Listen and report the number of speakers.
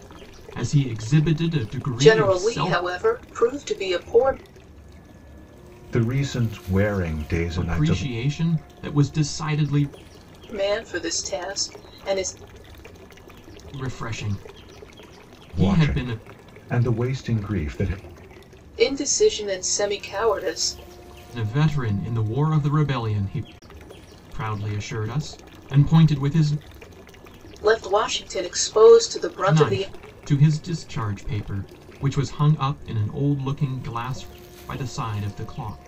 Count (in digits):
3